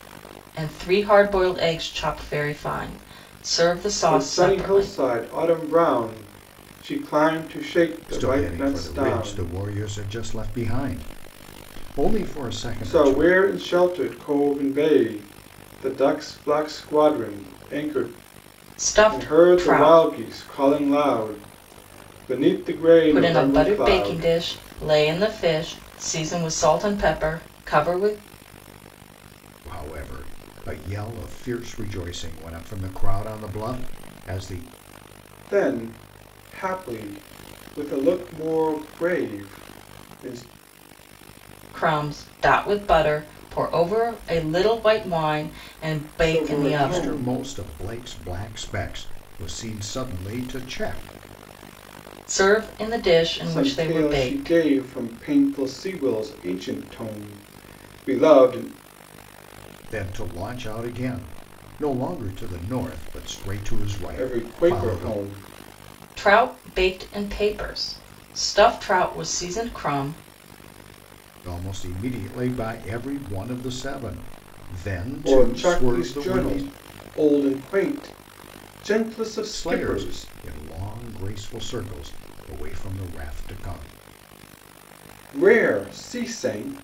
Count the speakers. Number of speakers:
3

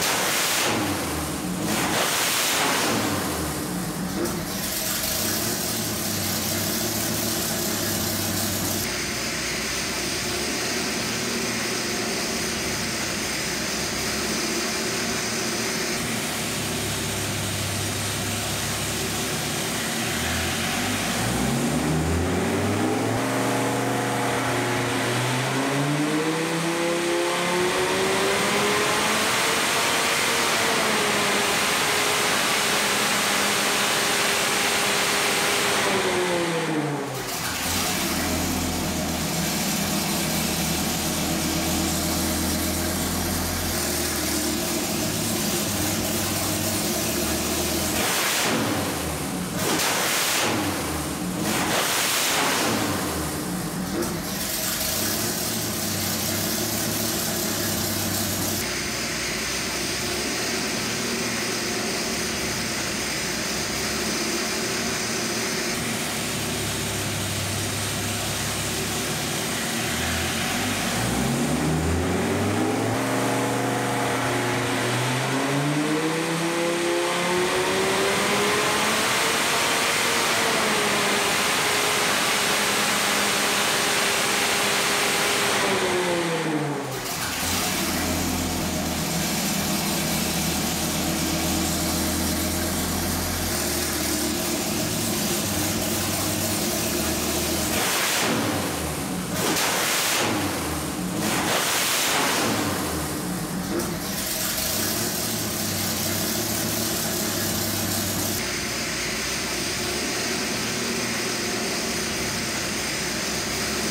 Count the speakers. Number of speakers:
0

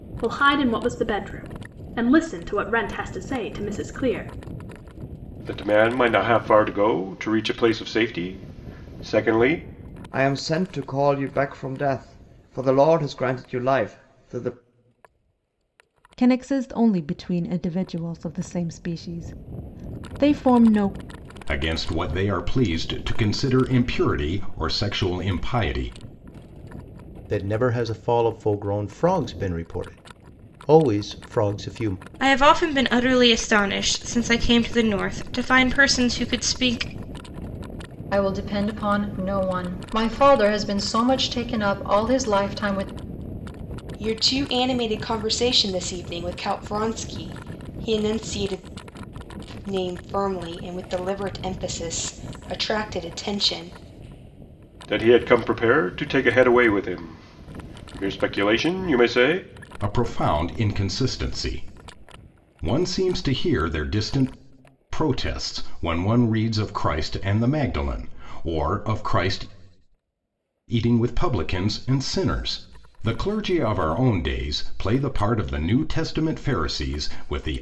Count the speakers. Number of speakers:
9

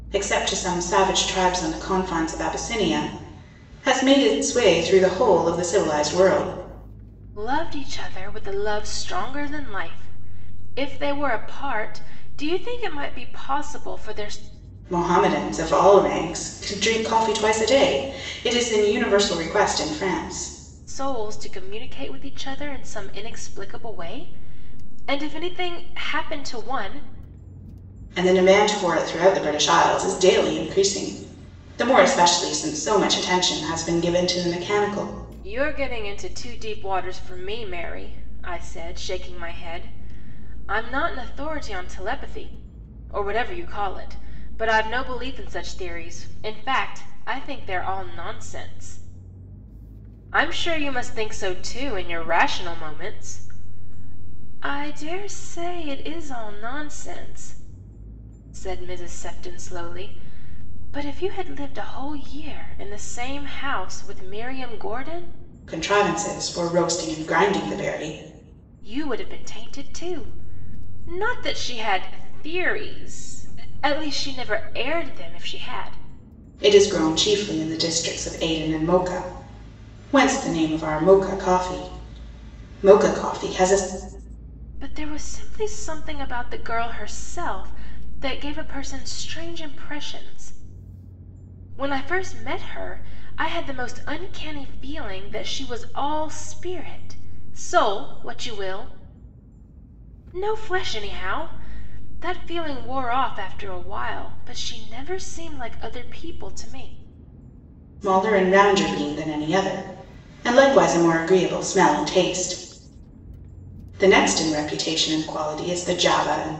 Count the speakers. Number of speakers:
2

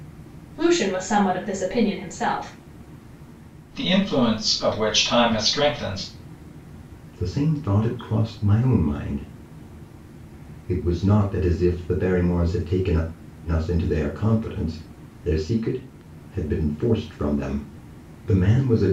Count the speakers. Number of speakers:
3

